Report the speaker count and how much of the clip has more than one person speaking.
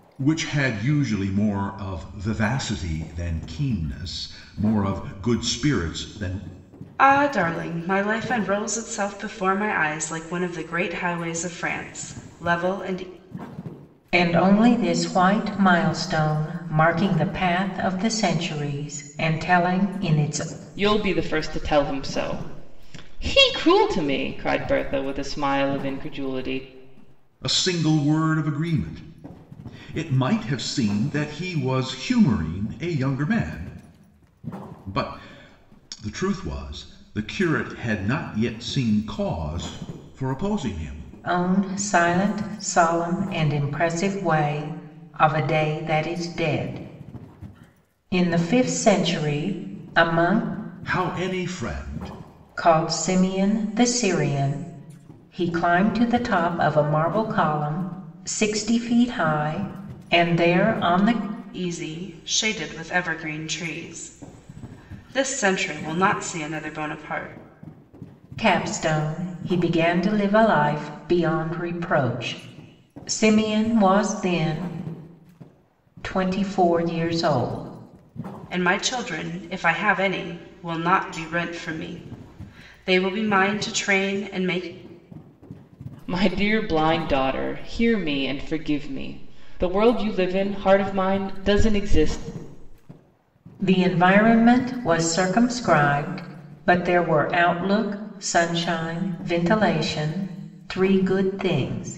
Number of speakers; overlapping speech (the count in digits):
4, no overlap